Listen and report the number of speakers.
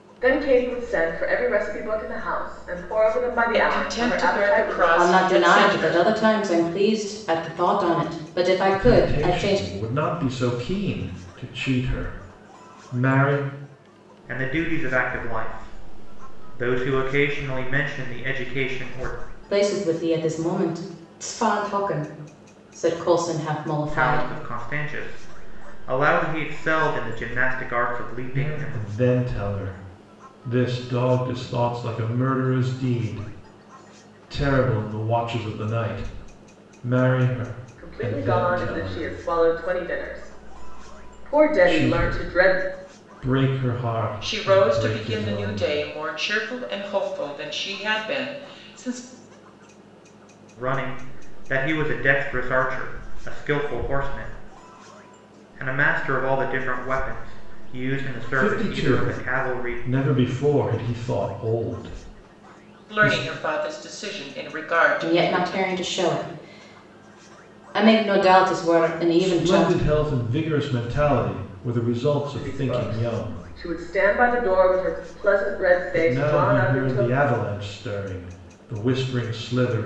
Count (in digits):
5